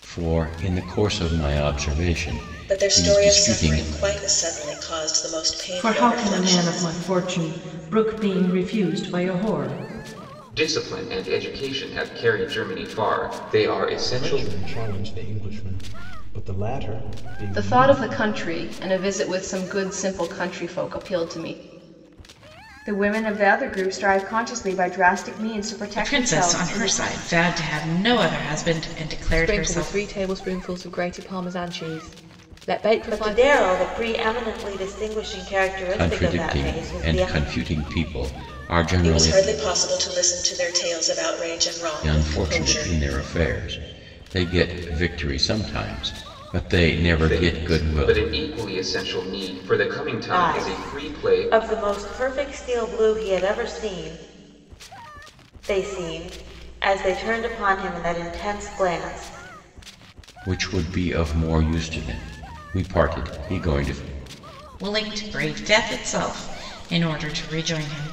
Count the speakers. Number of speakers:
10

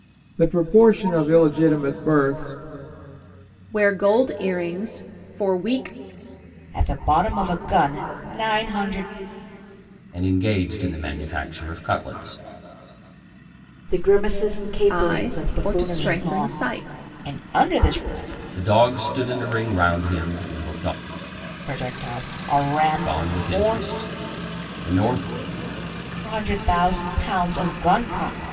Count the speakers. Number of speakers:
5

